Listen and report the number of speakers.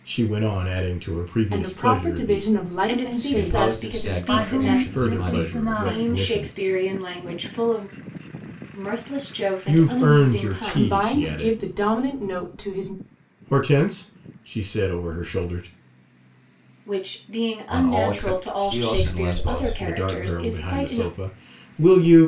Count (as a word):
five